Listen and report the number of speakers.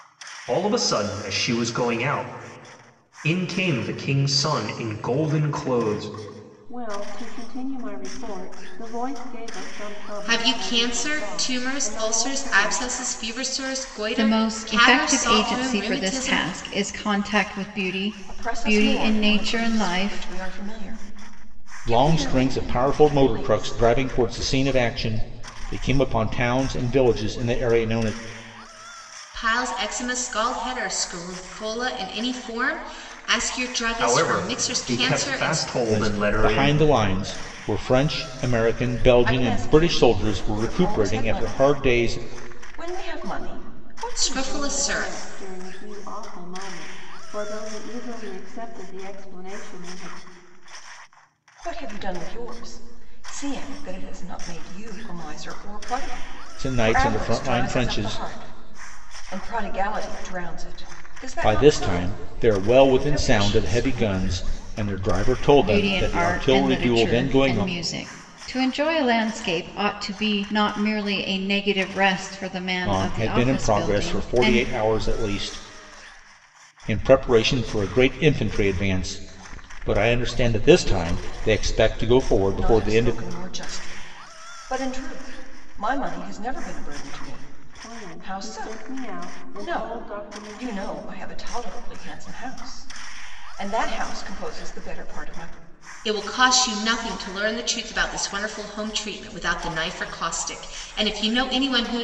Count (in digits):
6